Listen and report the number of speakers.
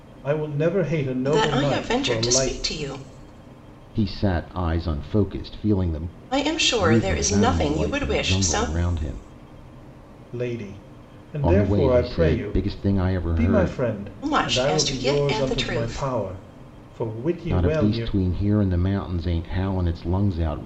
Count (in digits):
3